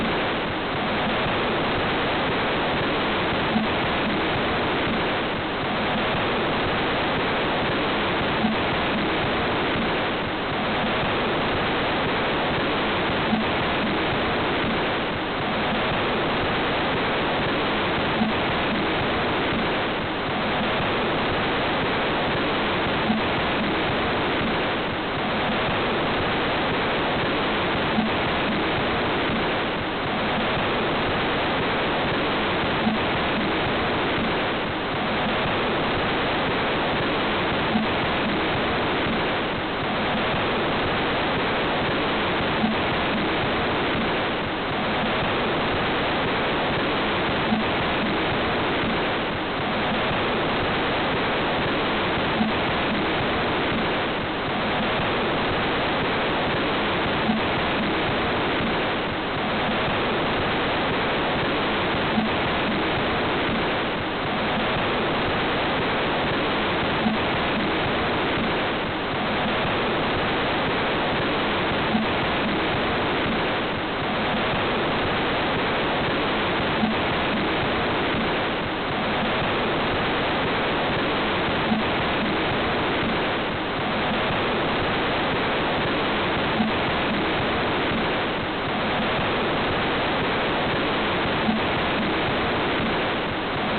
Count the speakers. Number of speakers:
zero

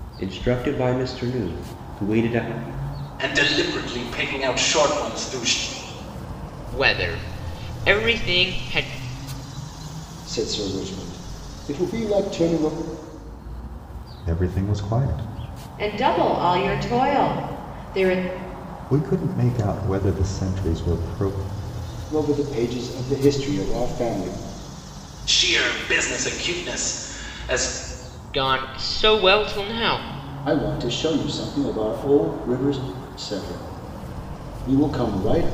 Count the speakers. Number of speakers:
six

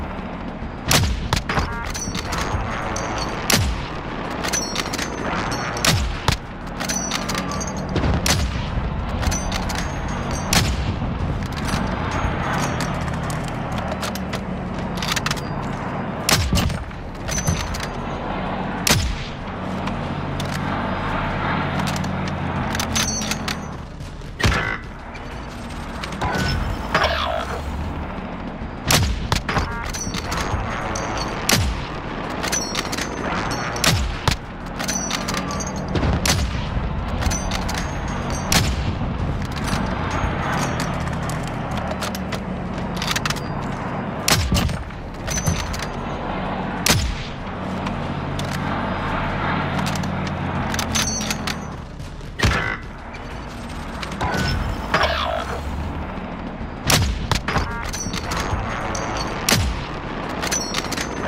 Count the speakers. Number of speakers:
zero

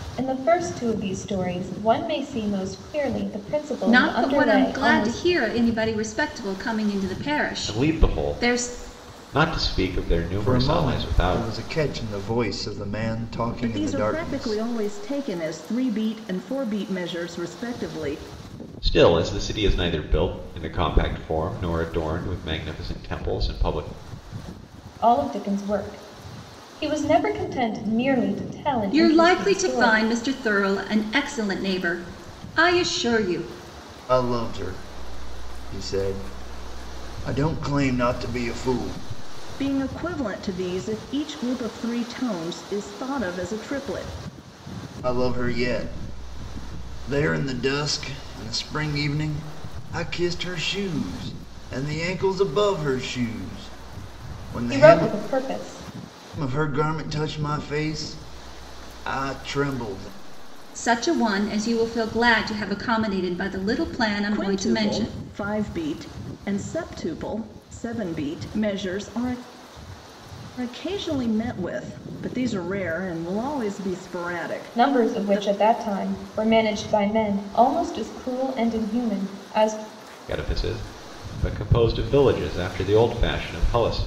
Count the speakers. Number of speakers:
five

